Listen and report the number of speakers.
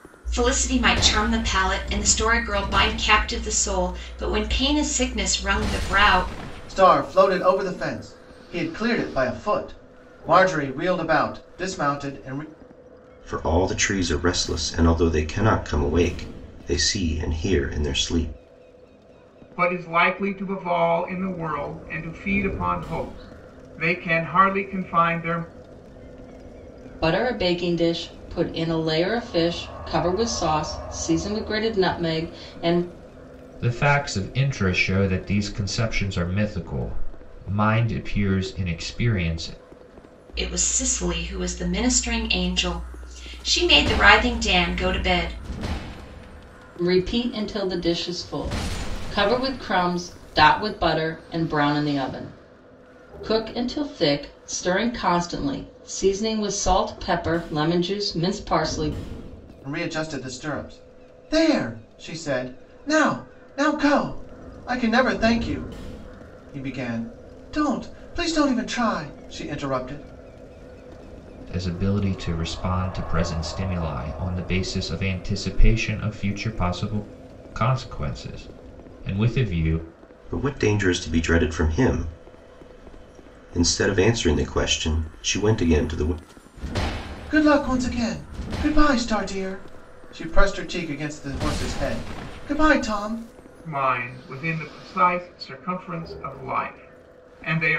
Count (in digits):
6